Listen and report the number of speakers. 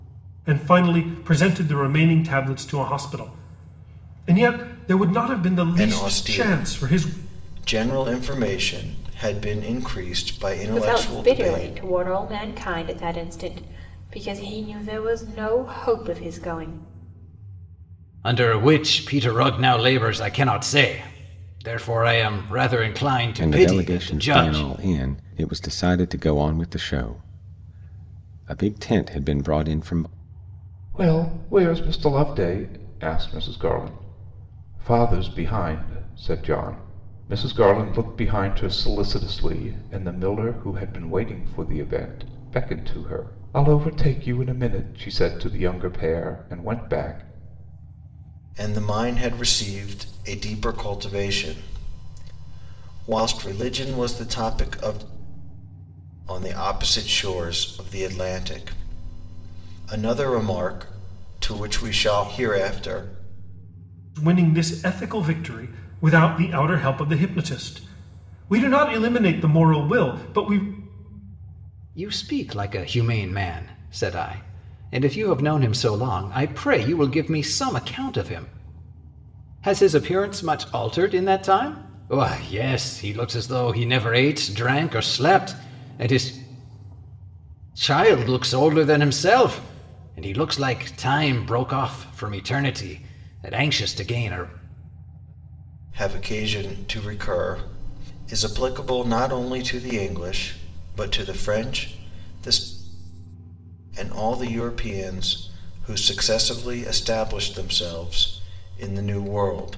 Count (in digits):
6